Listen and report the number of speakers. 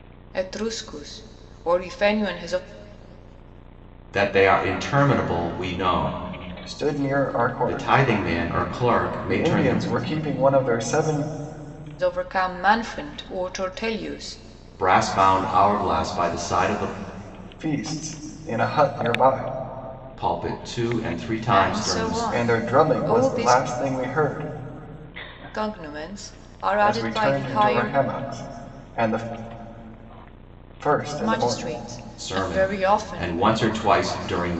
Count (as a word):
three